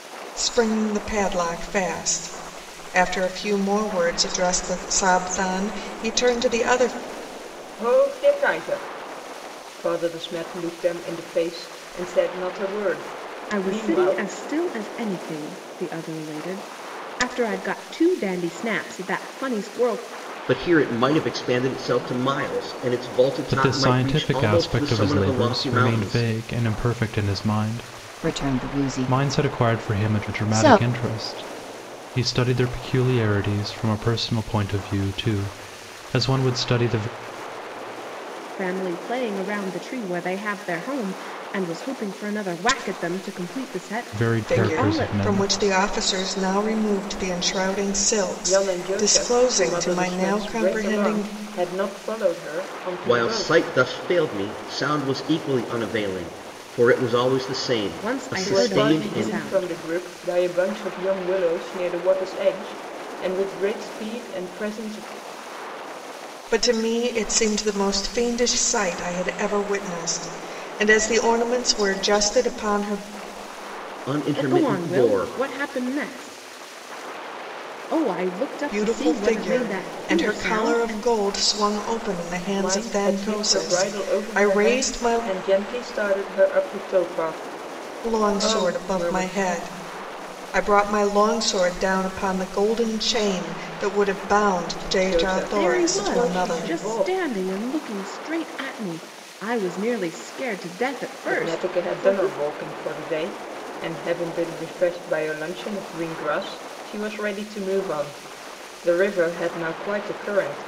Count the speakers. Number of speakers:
6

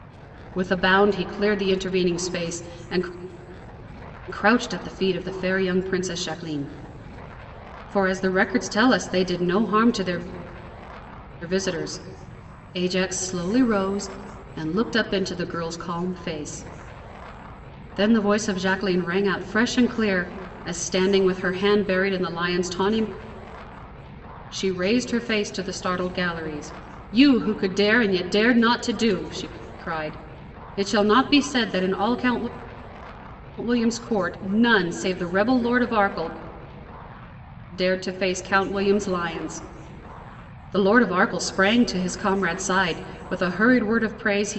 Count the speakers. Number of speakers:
1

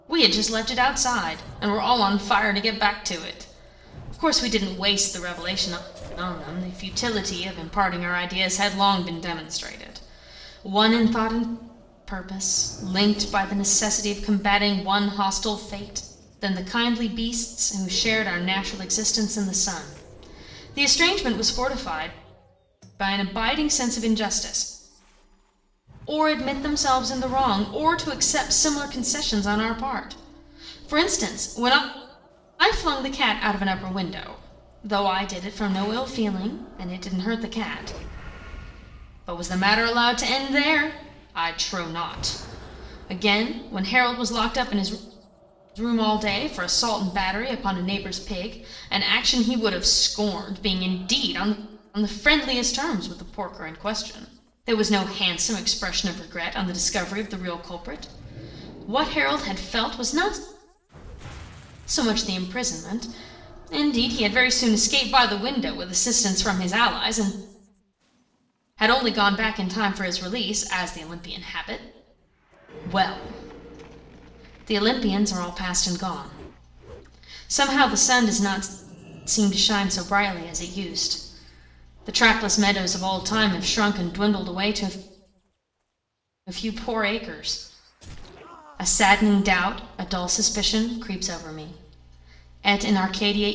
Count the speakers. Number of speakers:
1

